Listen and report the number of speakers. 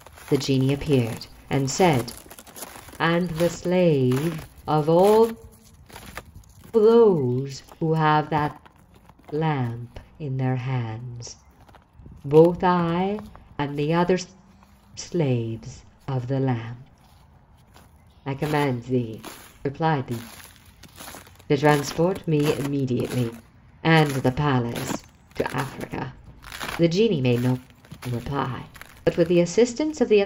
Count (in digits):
1